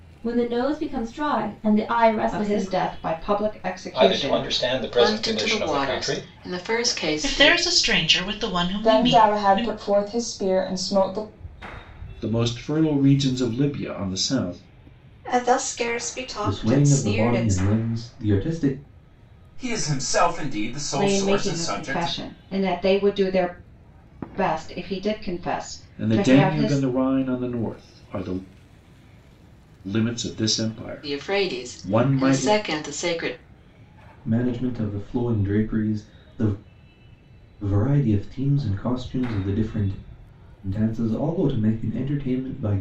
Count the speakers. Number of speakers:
10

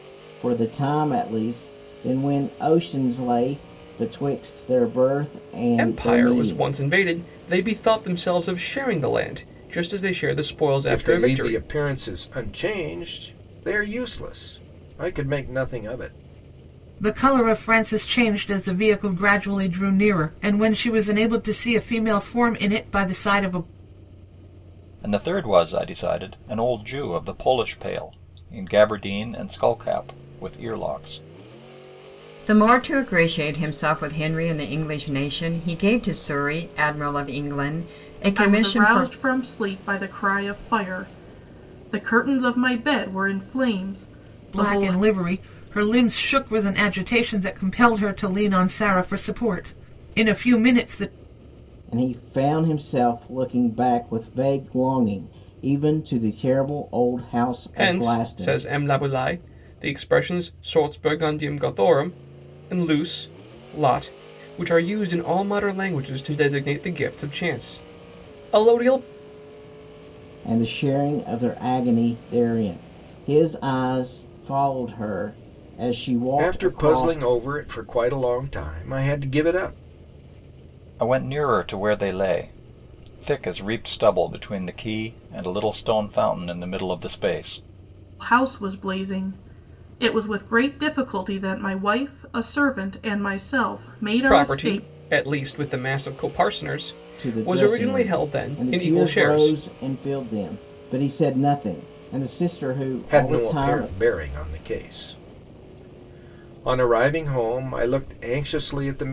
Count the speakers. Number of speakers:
7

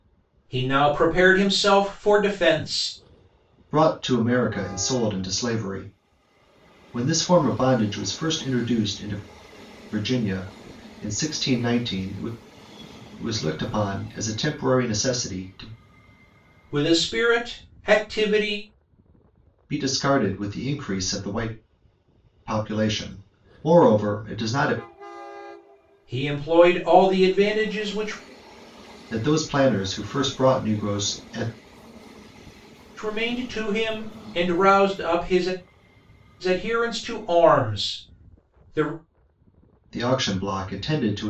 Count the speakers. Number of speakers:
2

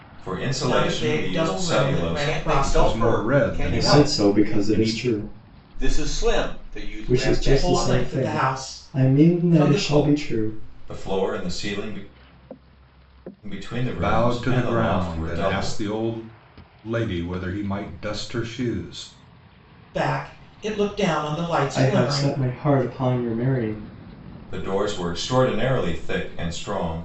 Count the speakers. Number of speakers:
5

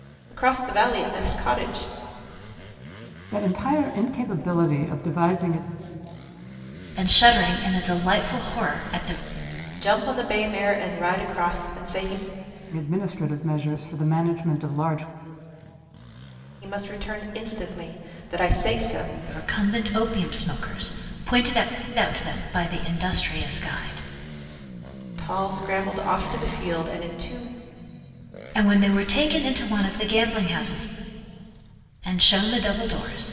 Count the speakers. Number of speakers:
3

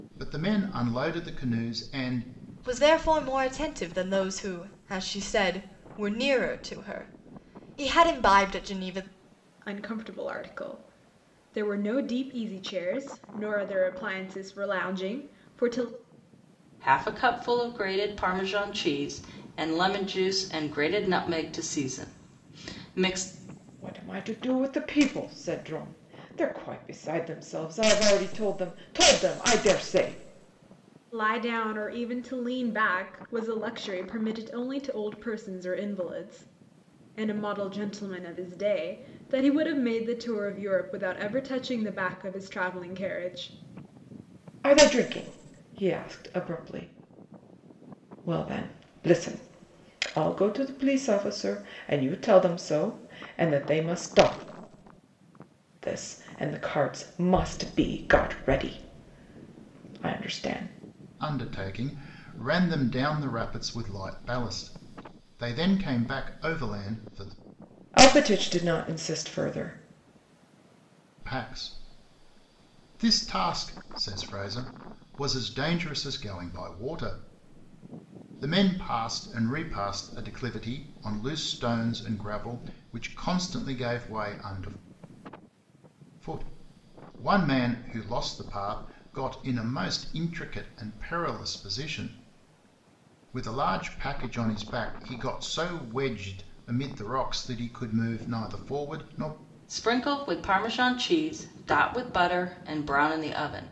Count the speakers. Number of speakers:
5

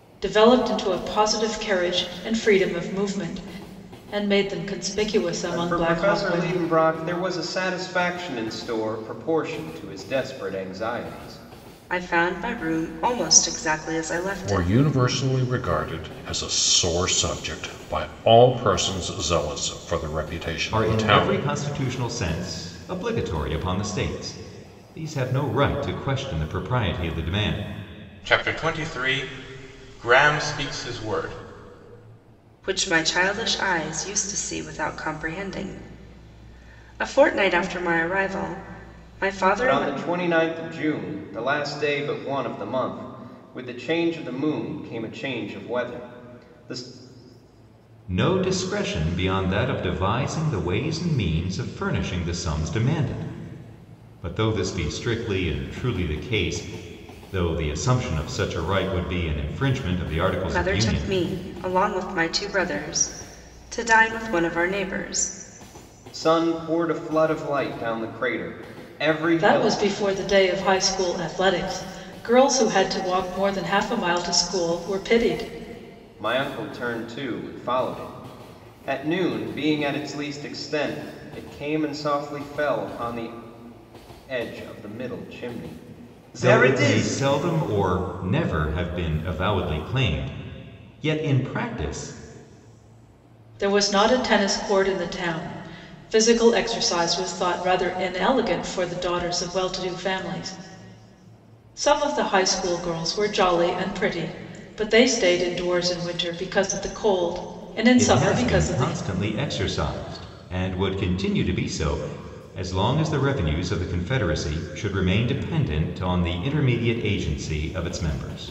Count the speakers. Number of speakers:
6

